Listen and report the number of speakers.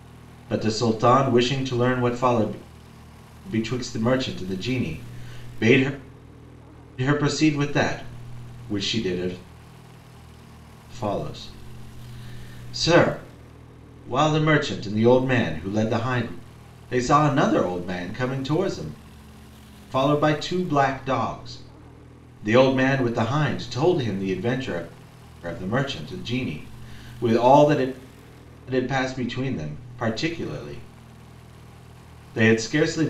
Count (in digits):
1